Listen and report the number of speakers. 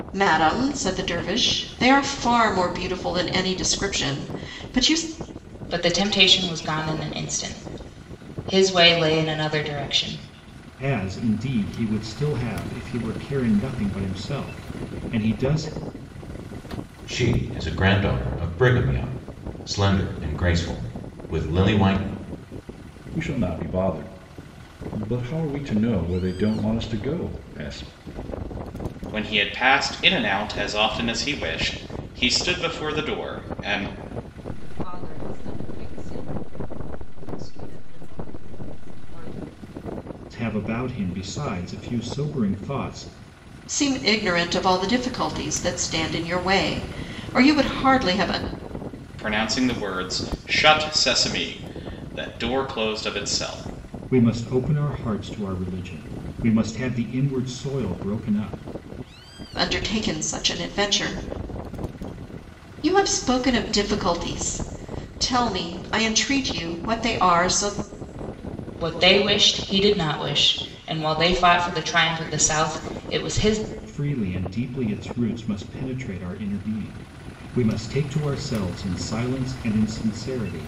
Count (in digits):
7